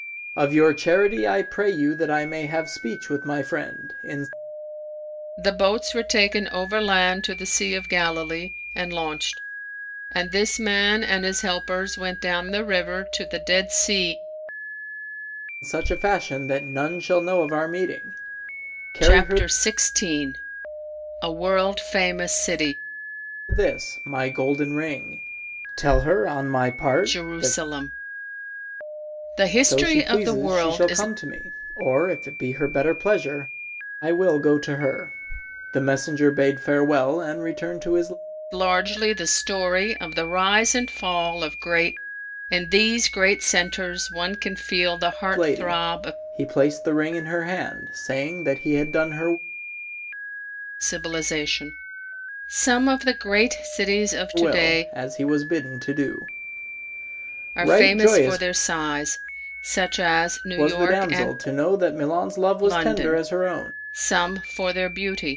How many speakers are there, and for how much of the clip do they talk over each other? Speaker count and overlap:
two, about 11%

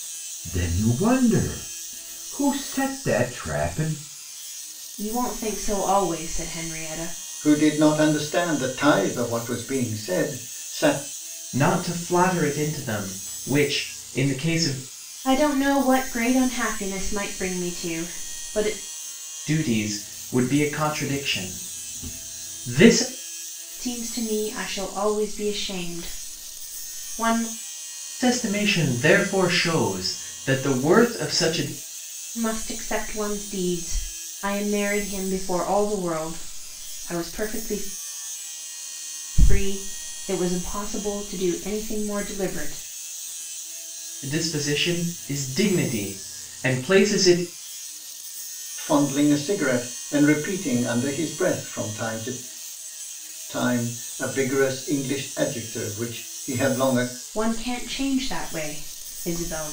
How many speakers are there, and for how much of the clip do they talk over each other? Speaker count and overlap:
four, no overlap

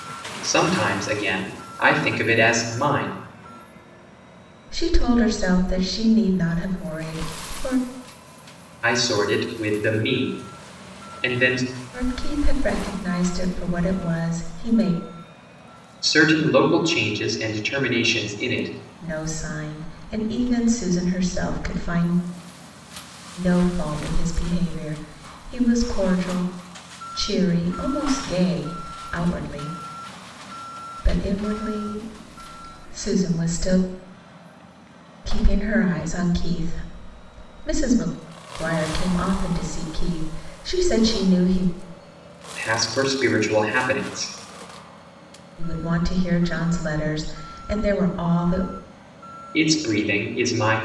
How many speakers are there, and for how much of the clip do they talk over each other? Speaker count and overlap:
two, no overlap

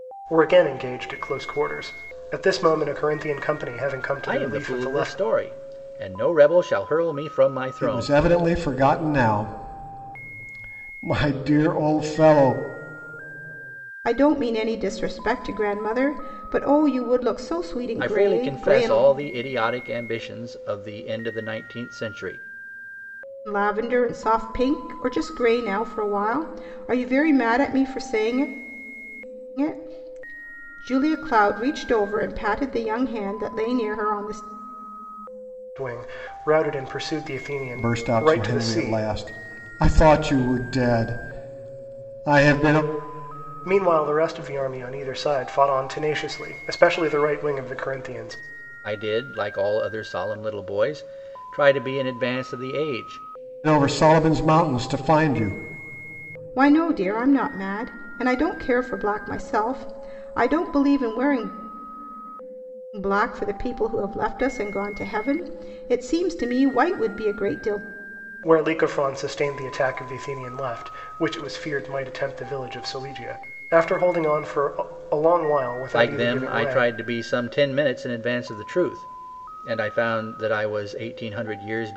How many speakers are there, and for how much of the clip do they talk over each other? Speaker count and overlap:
four, about 6%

